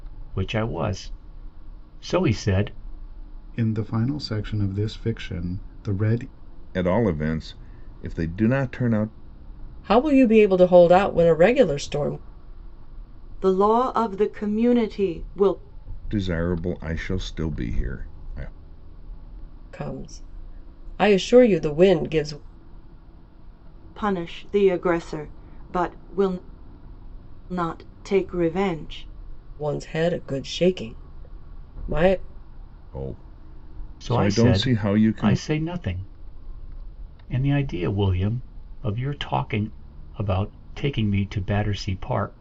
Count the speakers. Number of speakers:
five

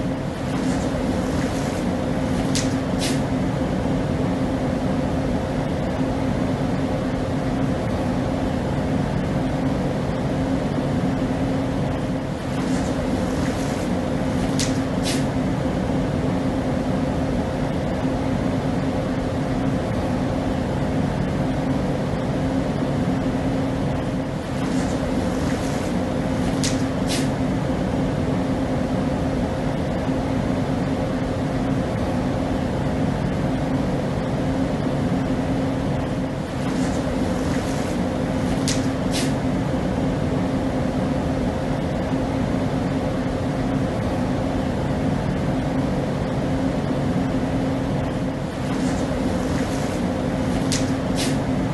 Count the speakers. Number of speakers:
zero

